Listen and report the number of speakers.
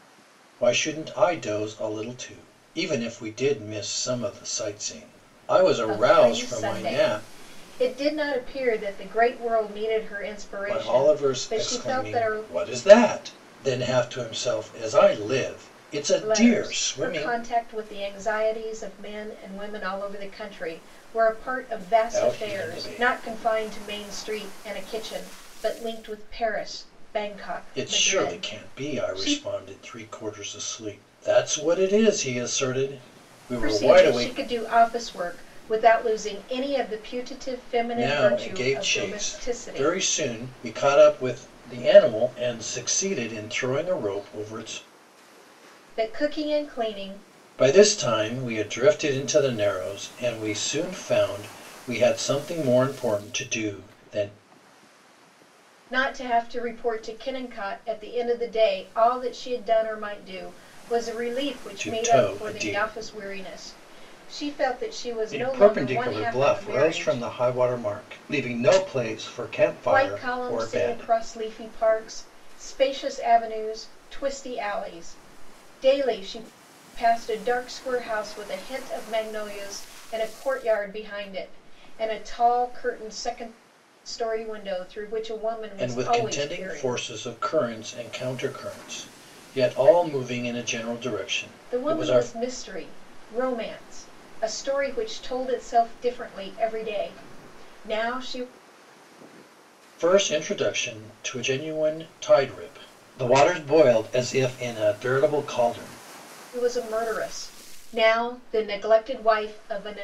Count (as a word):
two